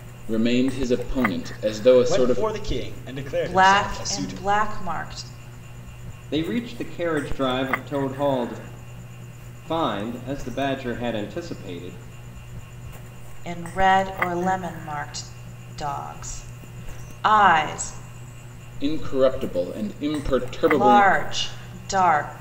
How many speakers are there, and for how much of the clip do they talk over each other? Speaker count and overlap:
4, about 9%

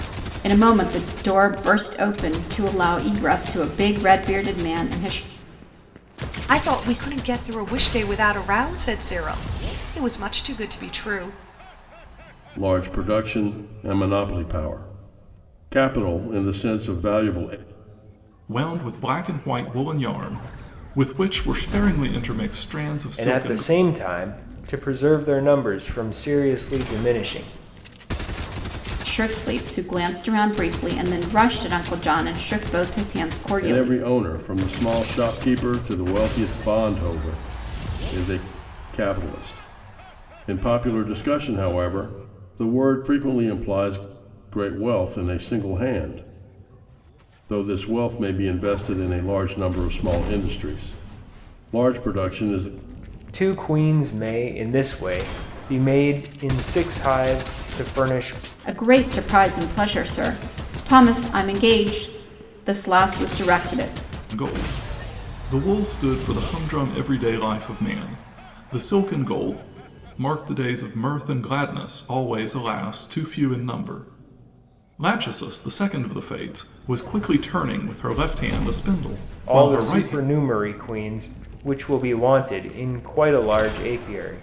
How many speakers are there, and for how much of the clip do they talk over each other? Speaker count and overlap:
5, about 2%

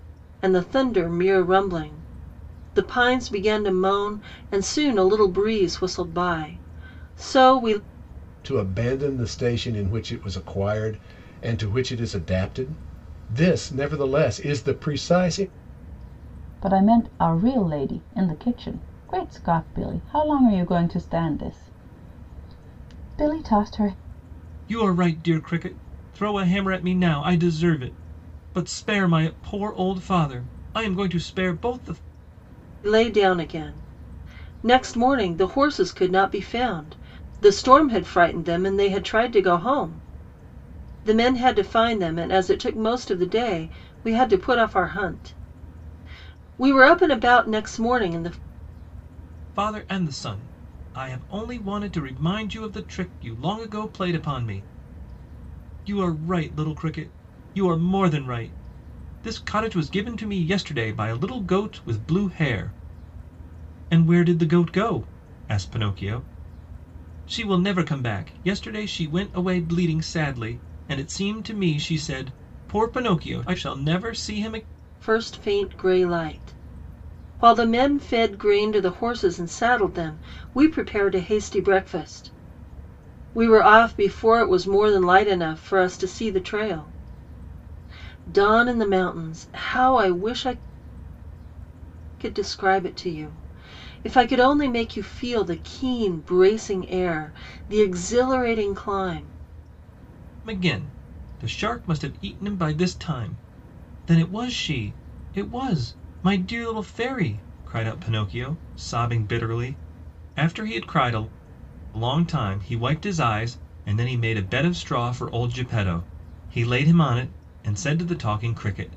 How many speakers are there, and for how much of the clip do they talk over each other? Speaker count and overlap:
4, no overlap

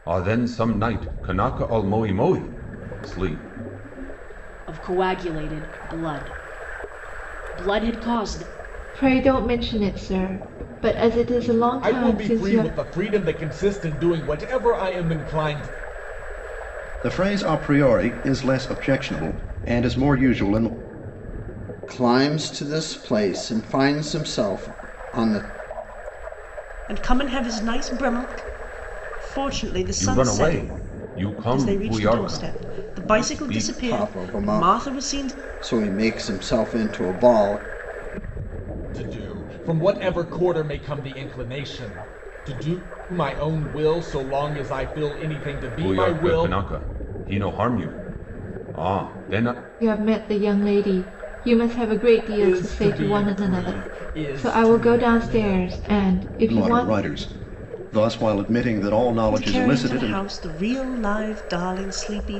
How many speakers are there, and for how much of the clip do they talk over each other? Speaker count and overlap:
7, about 18%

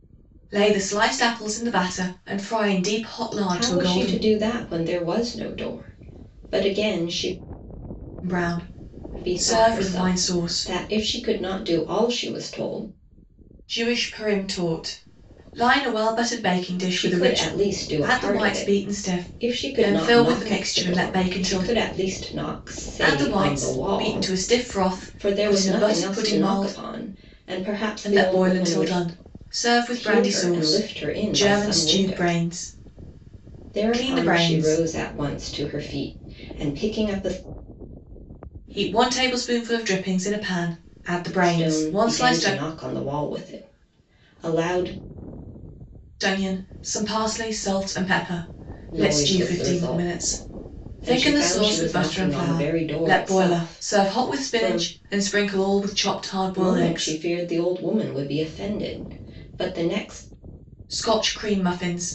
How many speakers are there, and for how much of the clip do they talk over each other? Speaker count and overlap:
2, about 33%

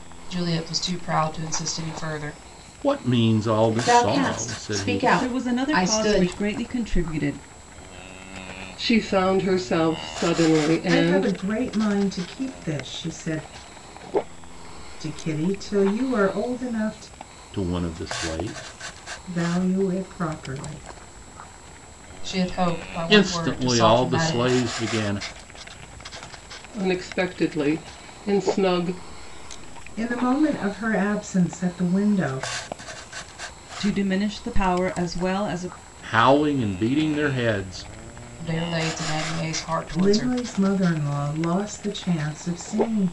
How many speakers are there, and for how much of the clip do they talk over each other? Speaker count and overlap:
6, about 11%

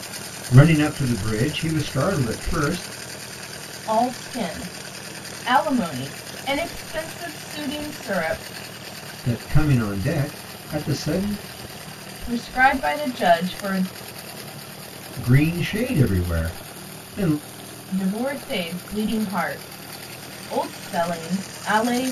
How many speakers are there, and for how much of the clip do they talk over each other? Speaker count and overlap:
2, no overlap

